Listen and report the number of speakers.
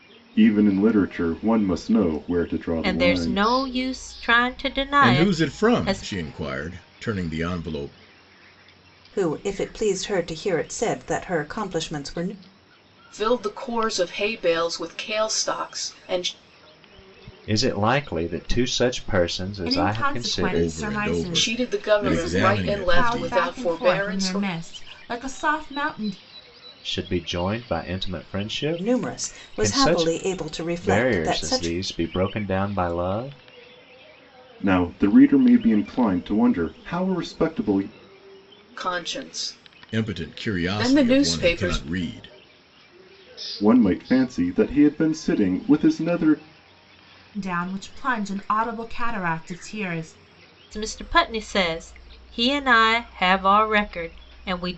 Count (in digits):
7